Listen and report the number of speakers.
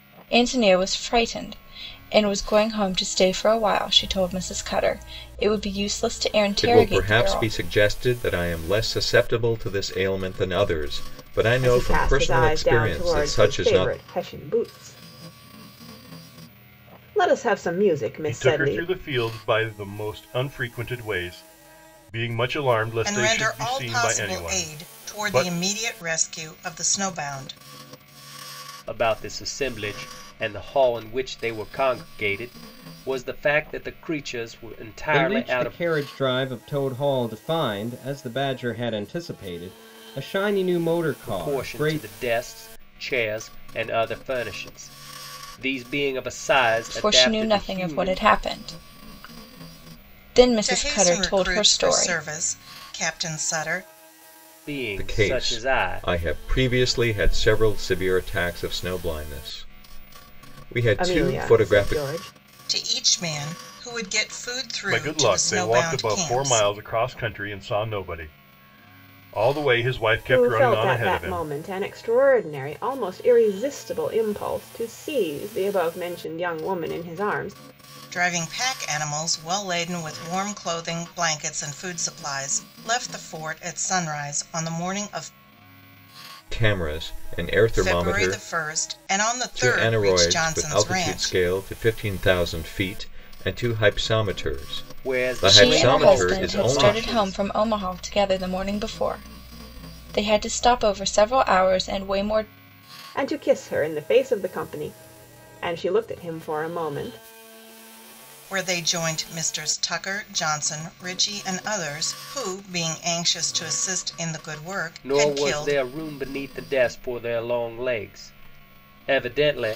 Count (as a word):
seven